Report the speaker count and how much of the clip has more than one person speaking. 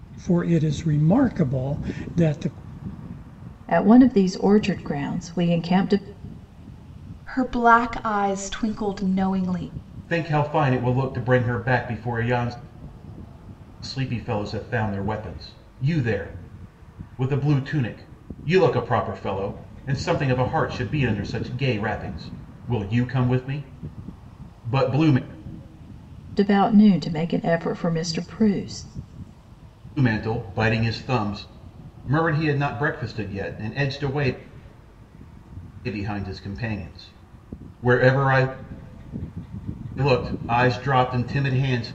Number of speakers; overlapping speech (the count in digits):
4, no overlap